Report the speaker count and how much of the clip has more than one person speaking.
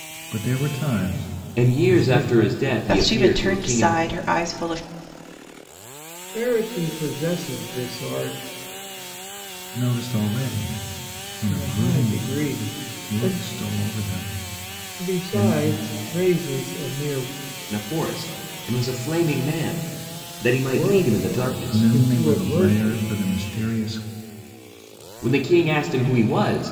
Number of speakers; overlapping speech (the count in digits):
4, about 23%